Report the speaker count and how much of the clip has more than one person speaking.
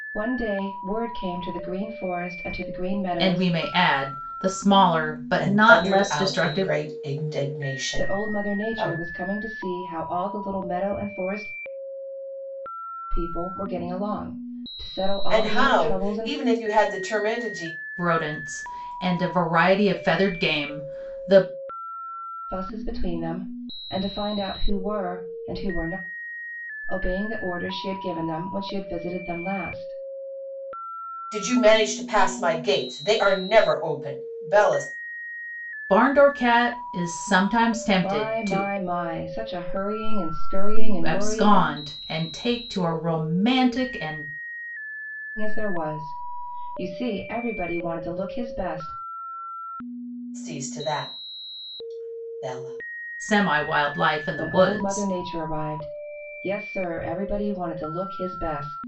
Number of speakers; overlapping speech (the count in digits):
3, about 11%